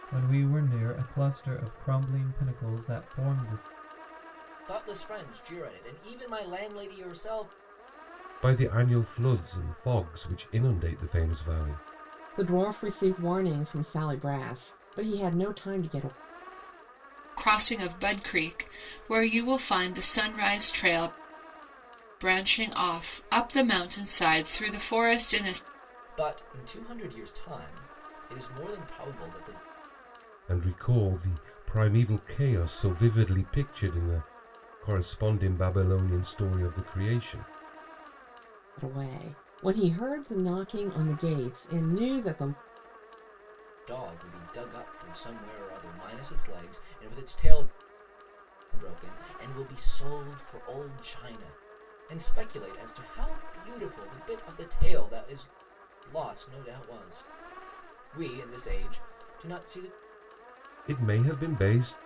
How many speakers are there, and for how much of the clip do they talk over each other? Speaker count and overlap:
5, no overlap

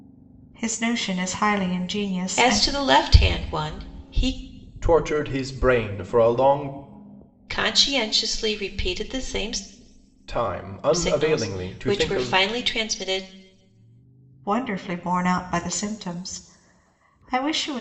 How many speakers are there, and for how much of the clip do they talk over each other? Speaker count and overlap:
3, about 10%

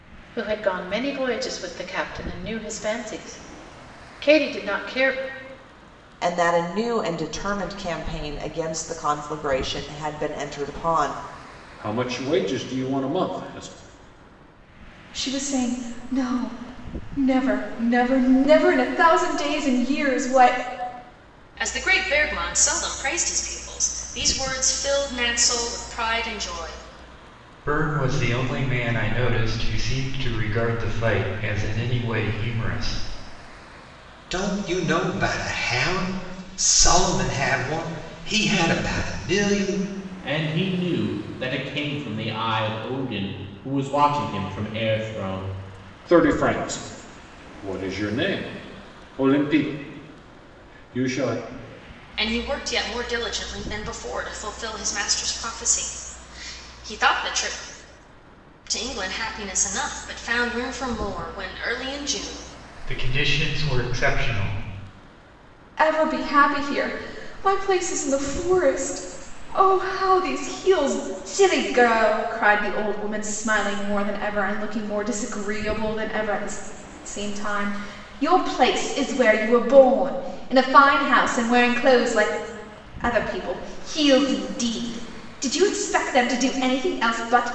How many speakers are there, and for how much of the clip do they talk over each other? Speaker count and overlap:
8, no overlap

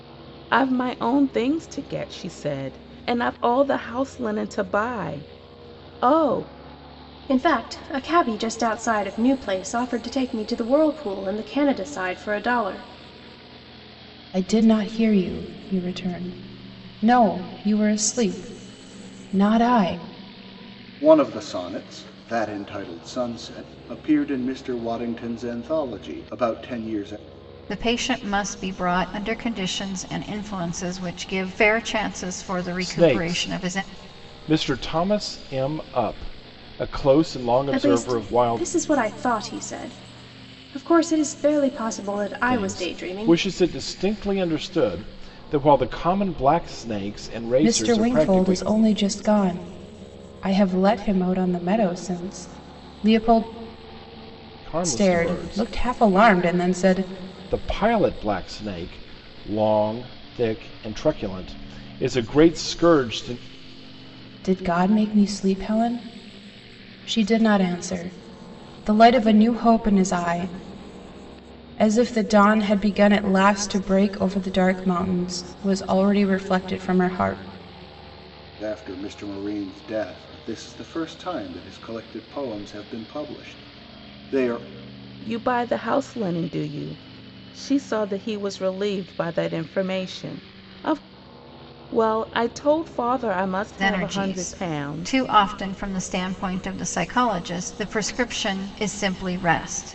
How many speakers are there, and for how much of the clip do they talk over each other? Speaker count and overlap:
6, about 6%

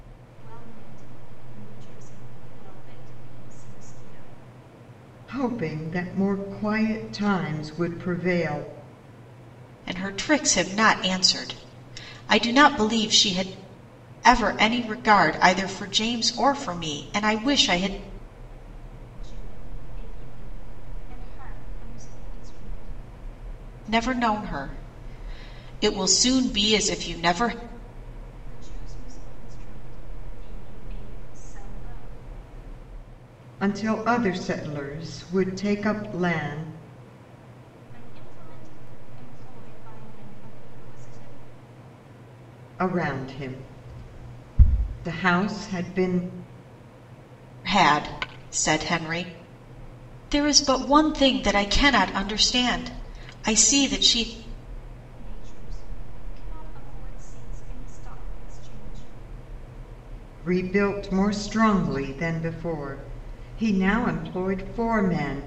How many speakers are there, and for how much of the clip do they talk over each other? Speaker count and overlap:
3, no overlap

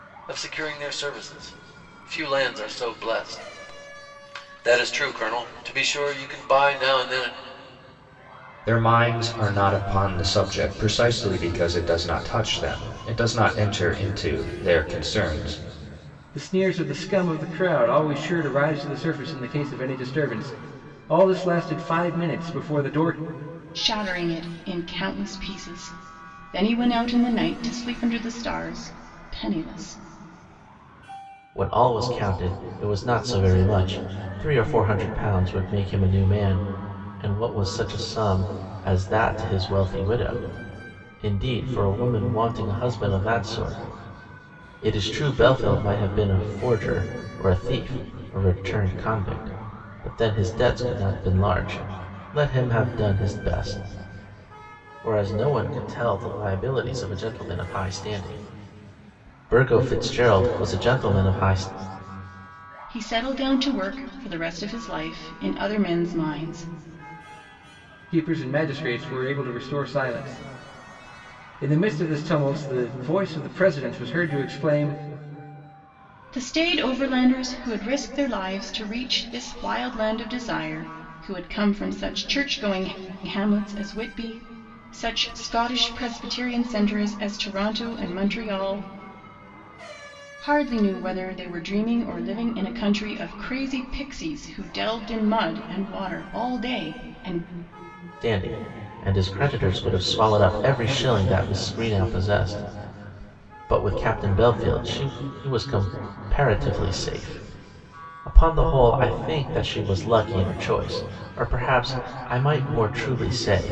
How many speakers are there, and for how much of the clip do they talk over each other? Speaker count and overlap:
5, no overlap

